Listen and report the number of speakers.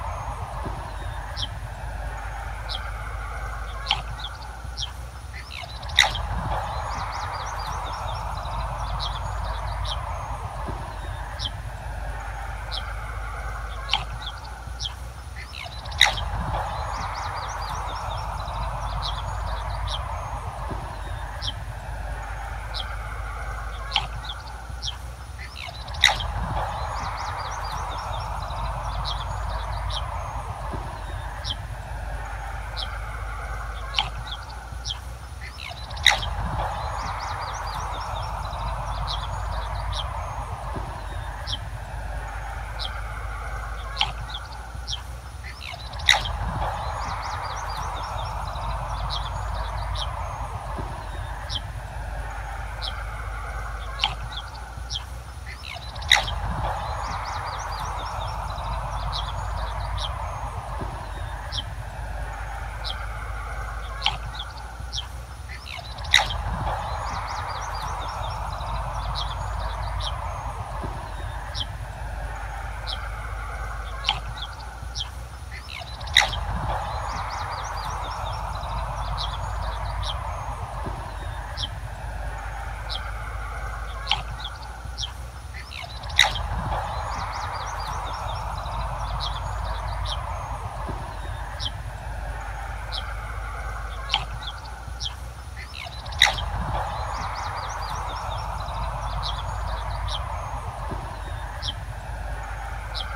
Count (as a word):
zero